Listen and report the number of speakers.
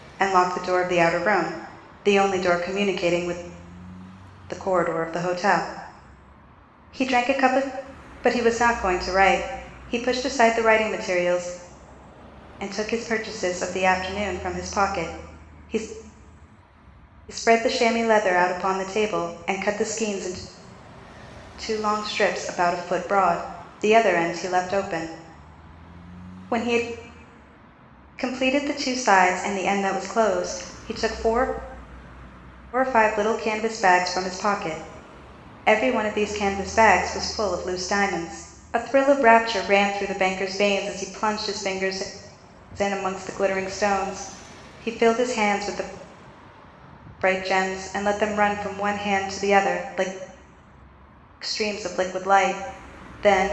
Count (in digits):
1